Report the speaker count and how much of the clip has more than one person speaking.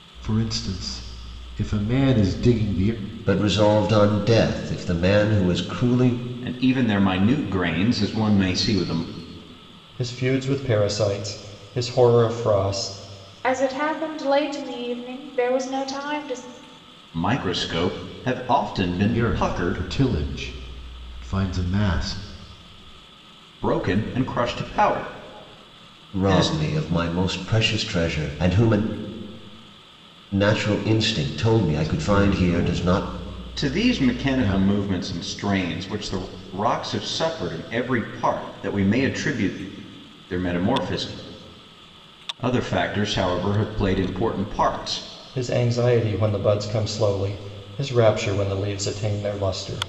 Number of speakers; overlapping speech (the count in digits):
5, about 7%